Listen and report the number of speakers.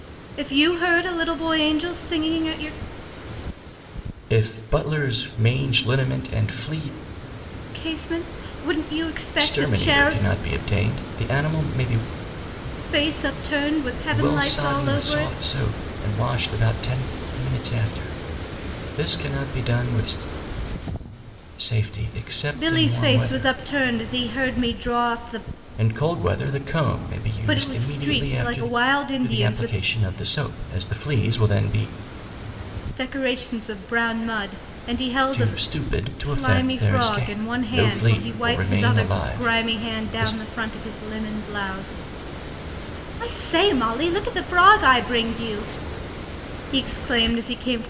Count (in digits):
2